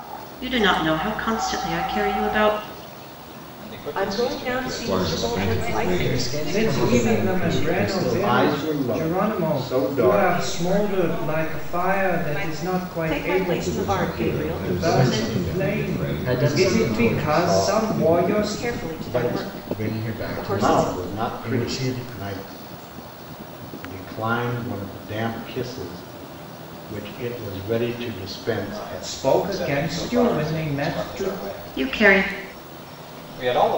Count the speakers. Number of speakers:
eight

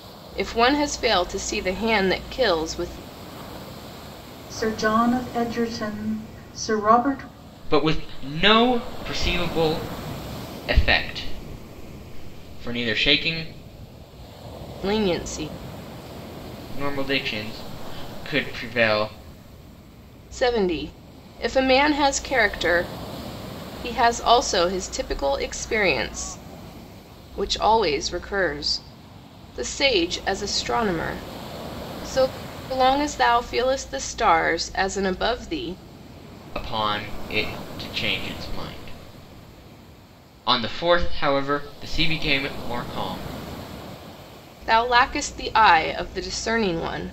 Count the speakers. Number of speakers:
three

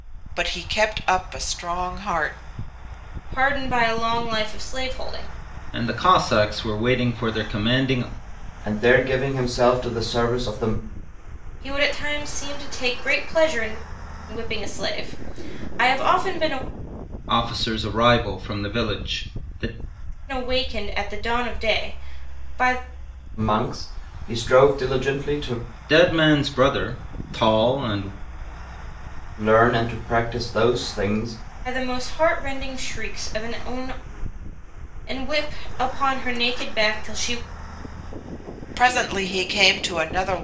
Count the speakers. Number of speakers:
four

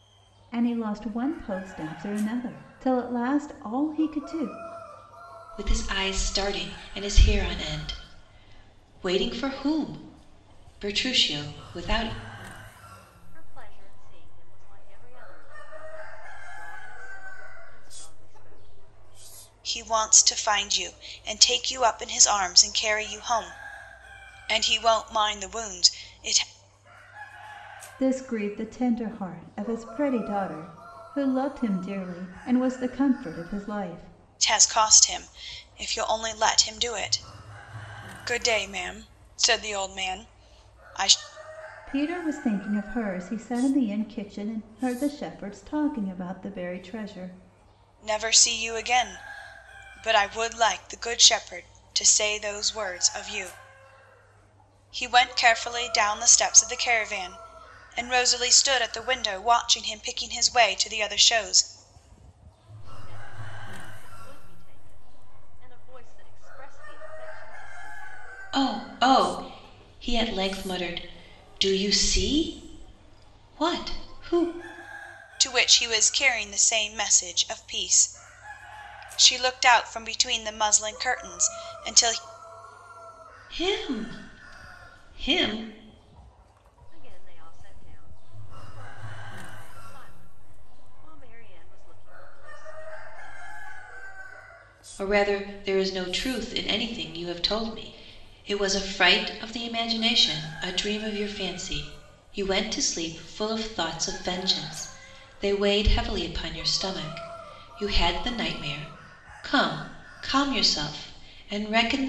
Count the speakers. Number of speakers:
four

